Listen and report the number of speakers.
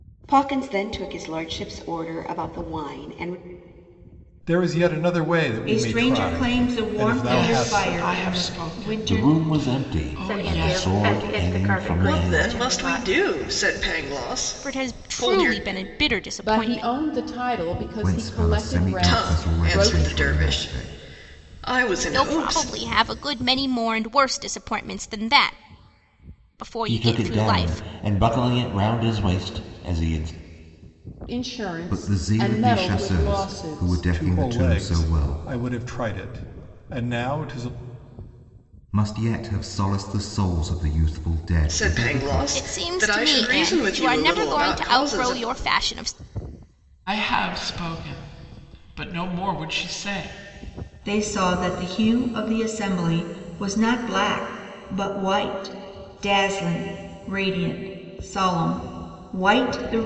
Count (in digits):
10